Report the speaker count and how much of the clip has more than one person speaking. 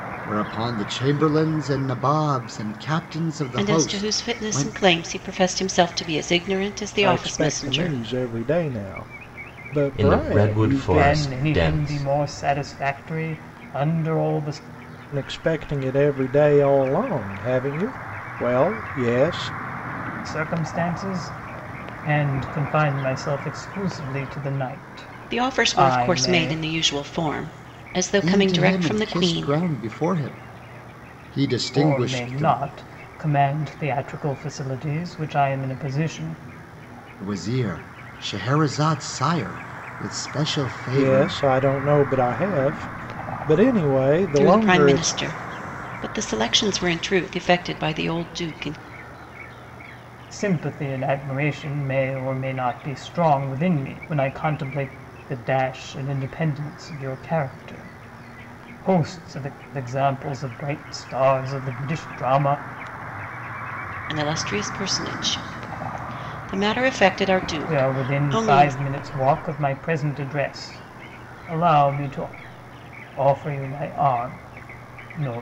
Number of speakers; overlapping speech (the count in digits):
5, about 14%